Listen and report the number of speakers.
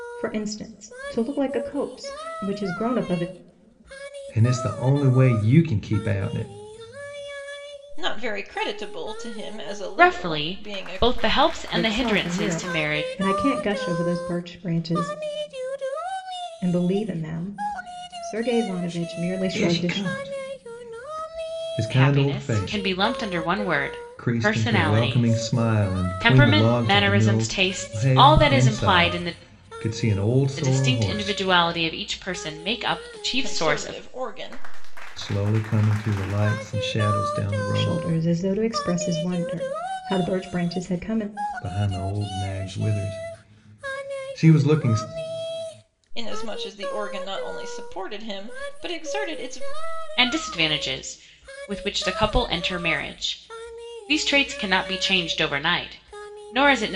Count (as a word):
four